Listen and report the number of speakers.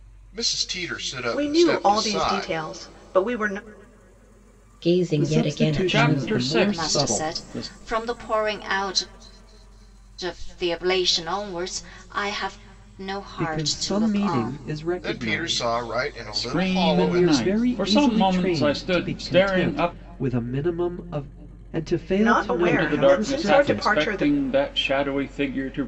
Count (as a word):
six